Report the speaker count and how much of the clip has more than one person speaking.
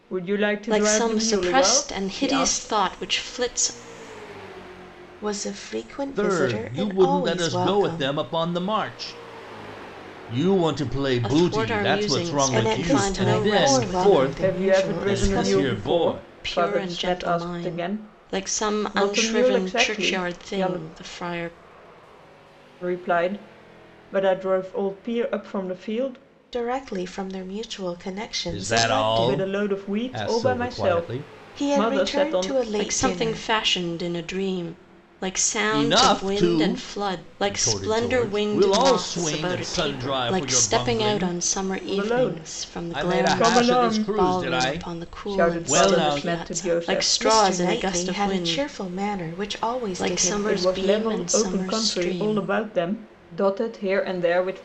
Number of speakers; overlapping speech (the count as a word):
four, about 60%